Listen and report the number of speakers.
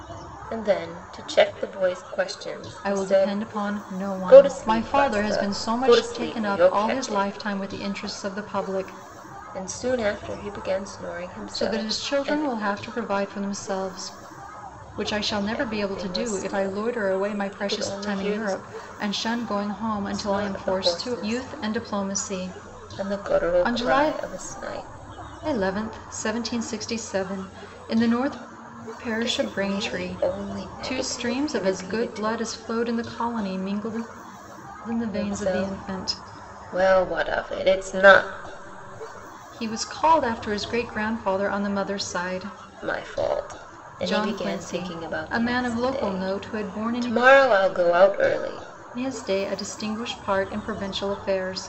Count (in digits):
2